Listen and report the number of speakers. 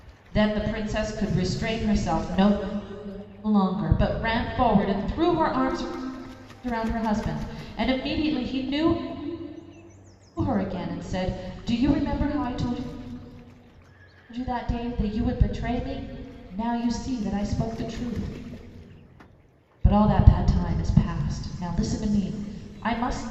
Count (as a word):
one